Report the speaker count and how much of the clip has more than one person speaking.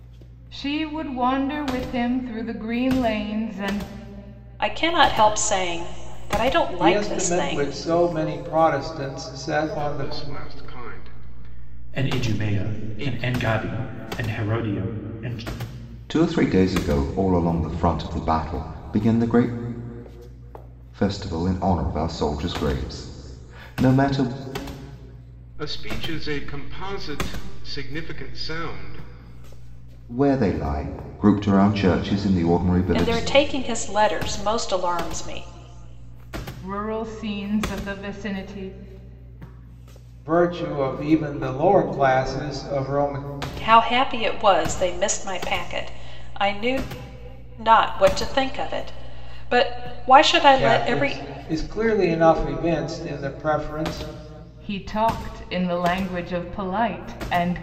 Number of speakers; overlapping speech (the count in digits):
6, about 7%